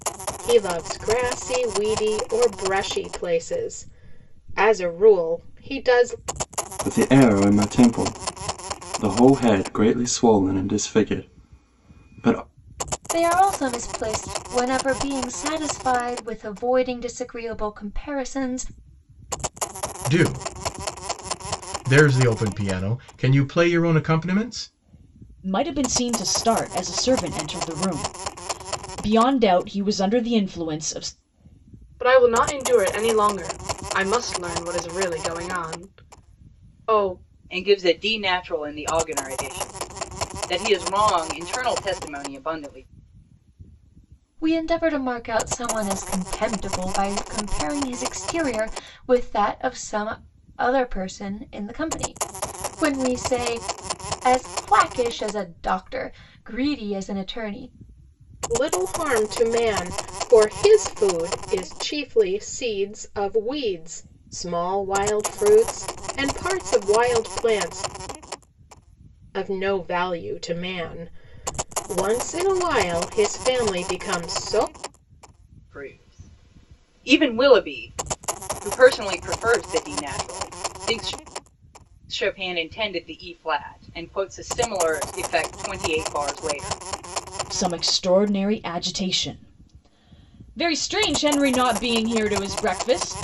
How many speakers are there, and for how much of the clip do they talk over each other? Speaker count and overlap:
seven, no overlap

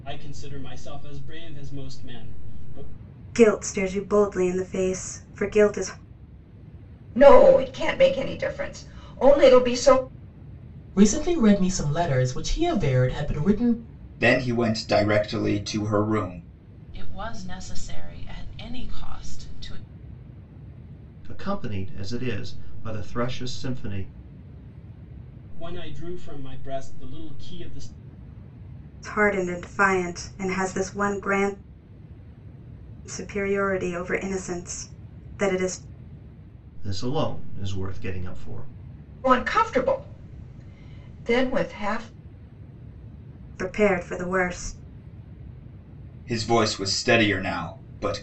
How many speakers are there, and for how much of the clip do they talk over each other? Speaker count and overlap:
seven, no overlap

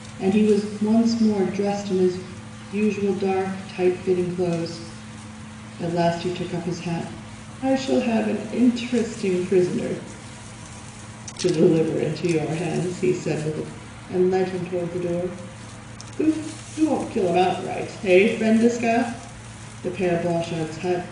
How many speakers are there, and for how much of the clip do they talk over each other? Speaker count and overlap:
one, no overlap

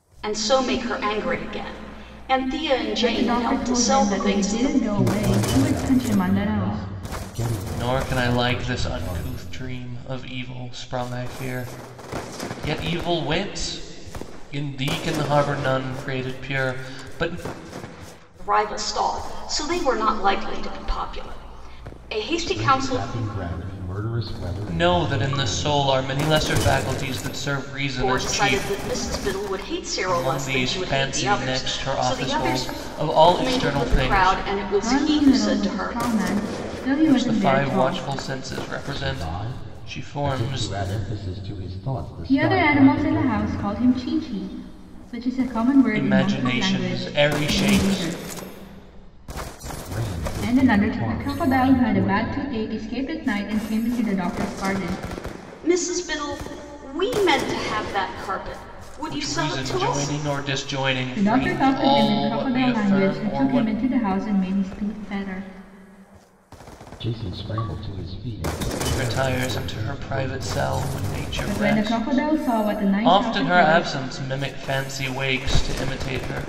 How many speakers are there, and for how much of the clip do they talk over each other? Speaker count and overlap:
four, about 42%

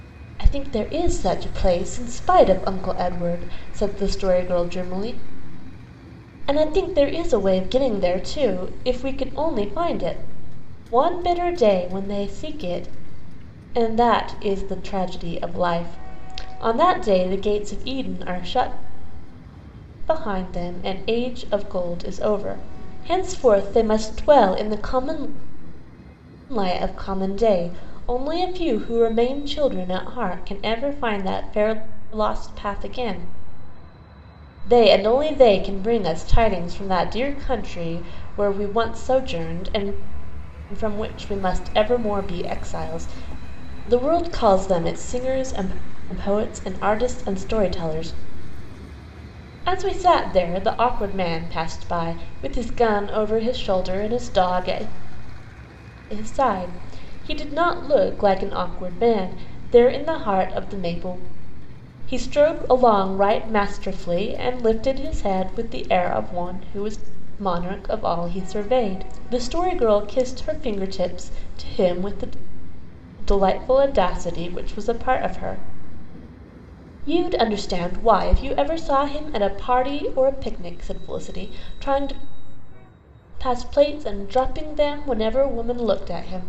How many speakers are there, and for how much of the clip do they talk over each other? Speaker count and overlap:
one, no overlap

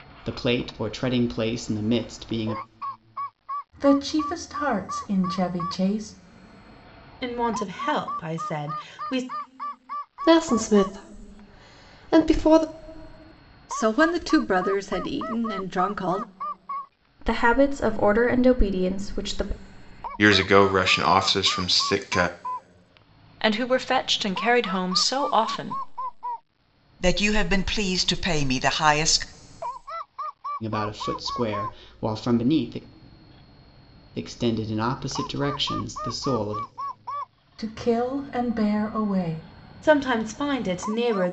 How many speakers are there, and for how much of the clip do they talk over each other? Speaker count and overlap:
nine, no overlap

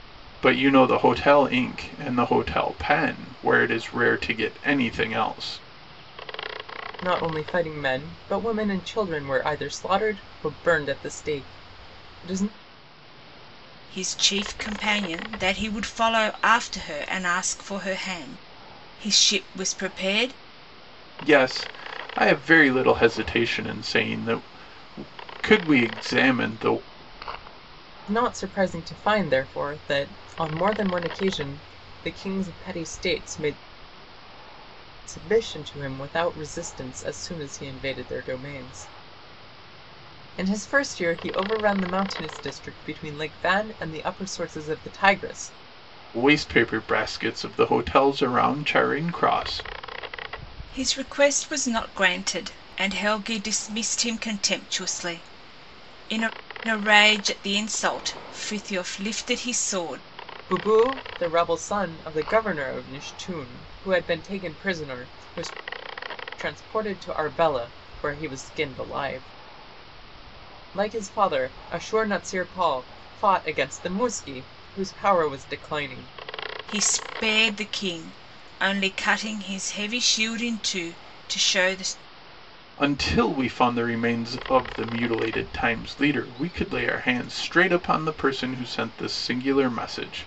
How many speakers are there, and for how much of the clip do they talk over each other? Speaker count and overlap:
three, no overlap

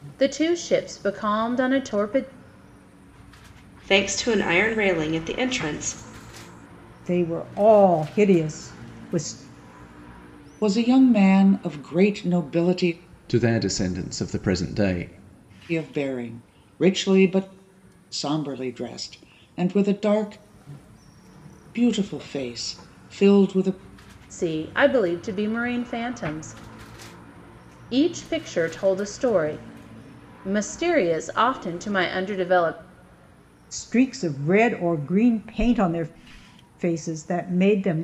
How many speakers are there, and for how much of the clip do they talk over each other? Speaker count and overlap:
five, no overlap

